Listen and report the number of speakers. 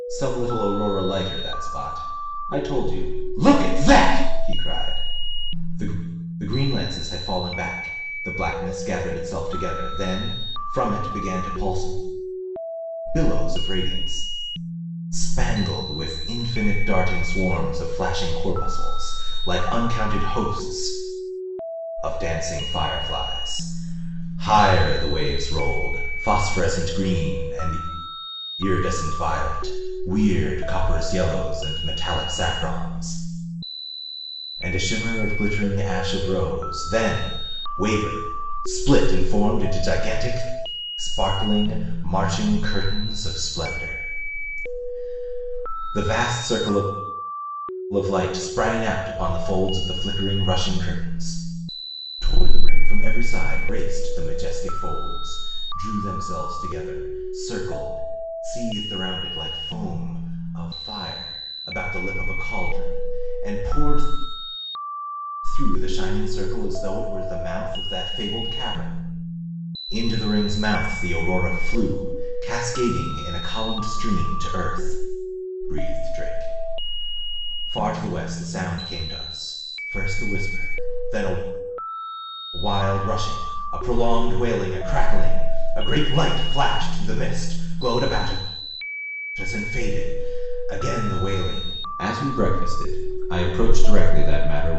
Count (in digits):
1